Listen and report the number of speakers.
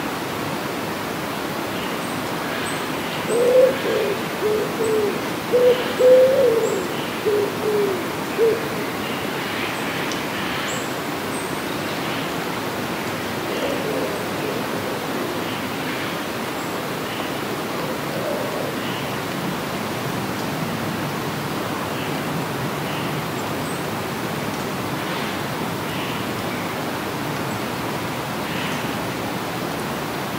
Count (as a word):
zero